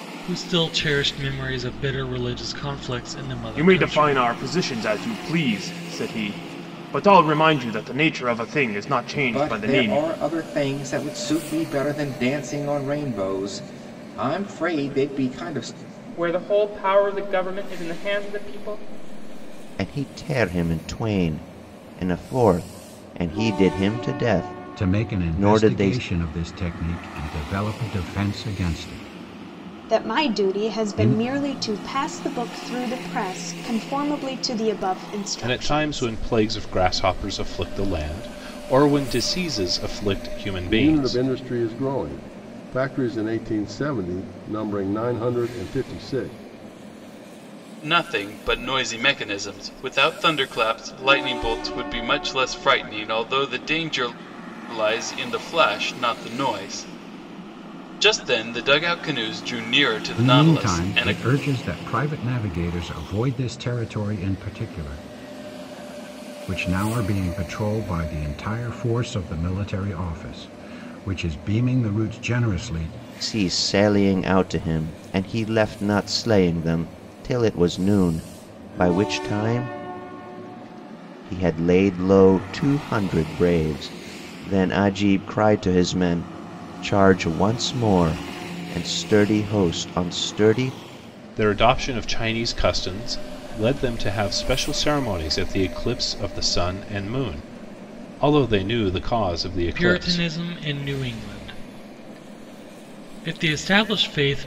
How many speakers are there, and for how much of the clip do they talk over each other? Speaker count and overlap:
ten, about 7%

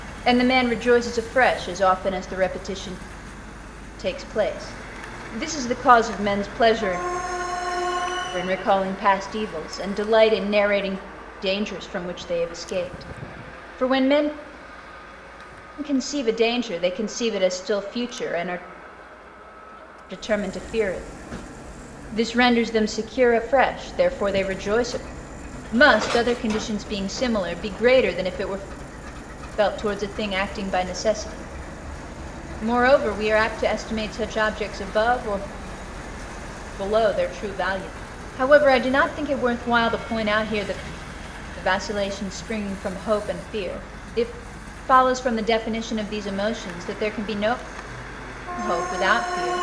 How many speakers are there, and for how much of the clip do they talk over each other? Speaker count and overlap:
one, no overlap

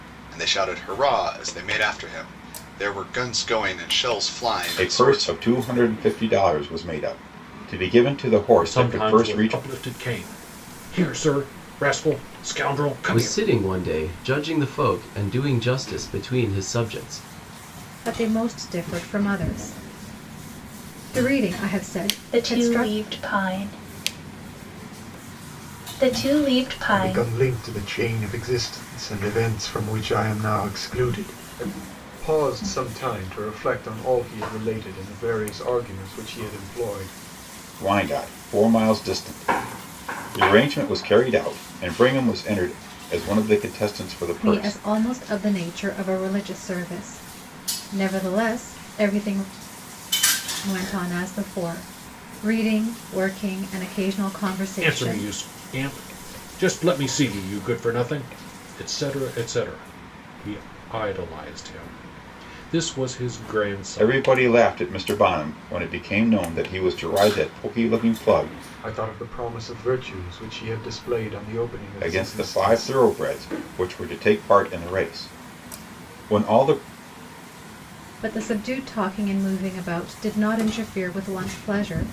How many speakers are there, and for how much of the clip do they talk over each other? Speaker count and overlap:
seven, about 7%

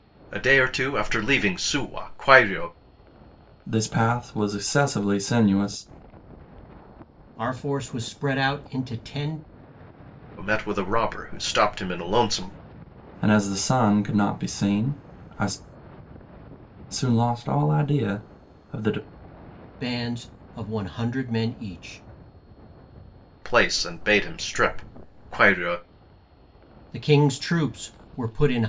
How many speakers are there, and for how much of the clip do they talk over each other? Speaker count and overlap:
three, no overlap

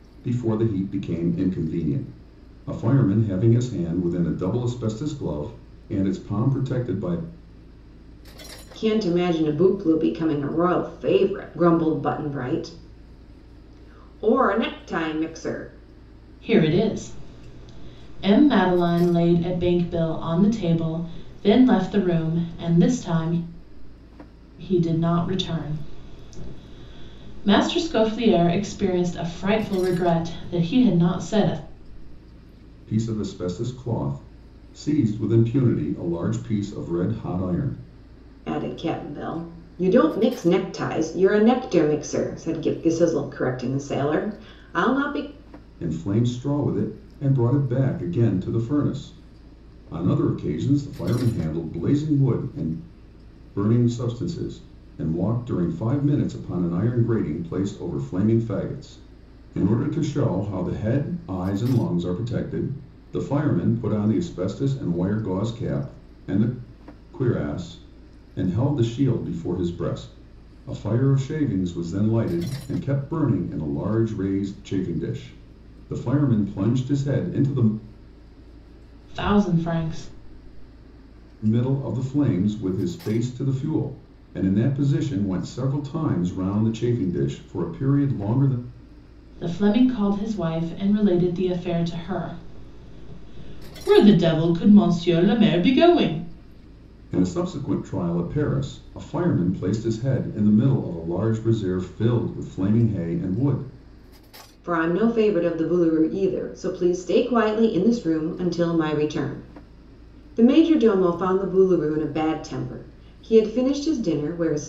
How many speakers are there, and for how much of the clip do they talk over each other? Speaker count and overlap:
three, no overlap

